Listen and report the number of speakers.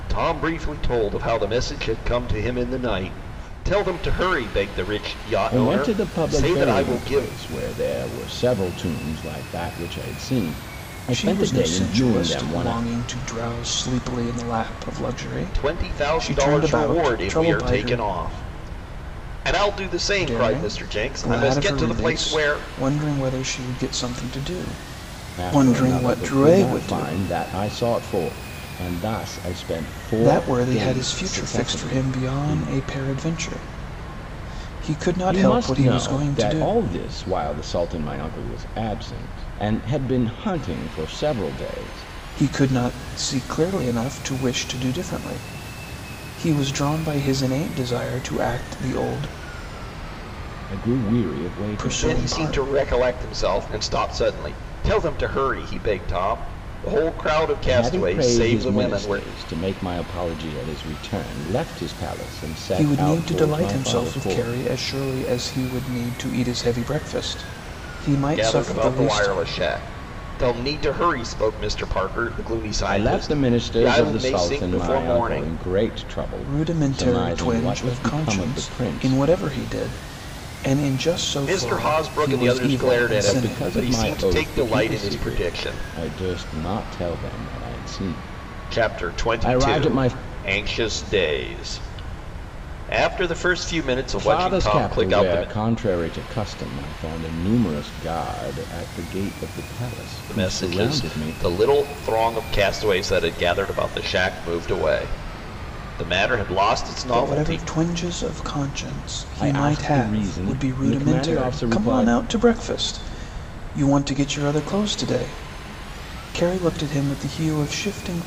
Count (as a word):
three